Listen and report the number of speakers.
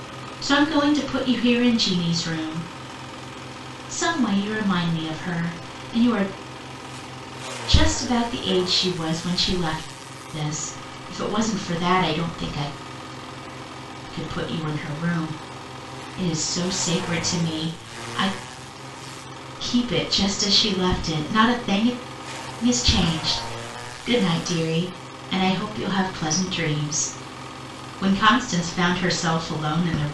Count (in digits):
1